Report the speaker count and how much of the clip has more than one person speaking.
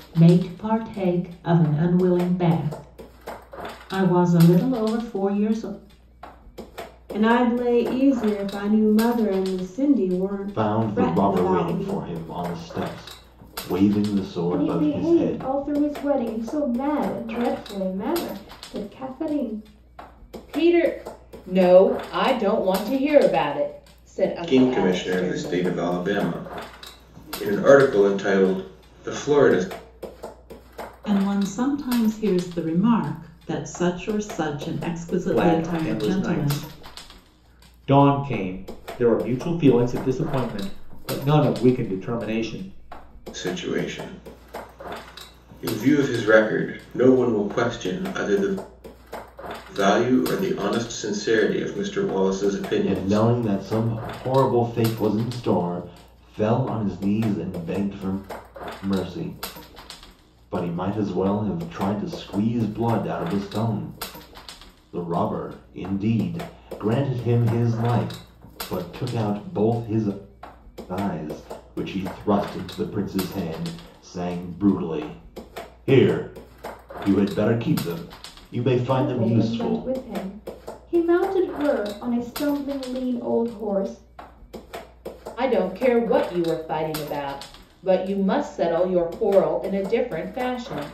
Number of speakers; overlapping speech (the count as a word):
eight, about 7%